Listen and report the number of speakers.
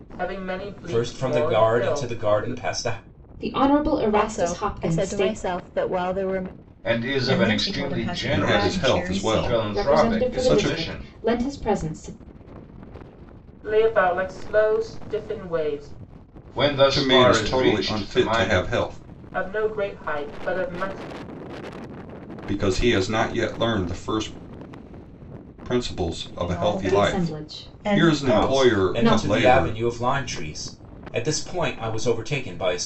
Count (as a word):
seven